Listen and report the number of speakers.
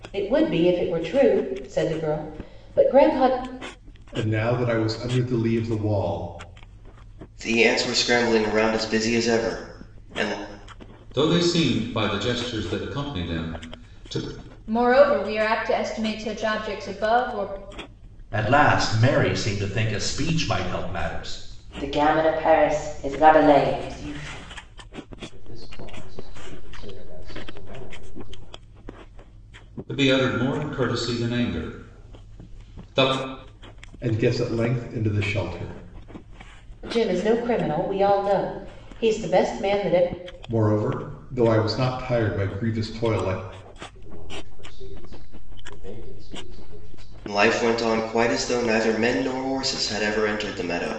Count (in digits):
8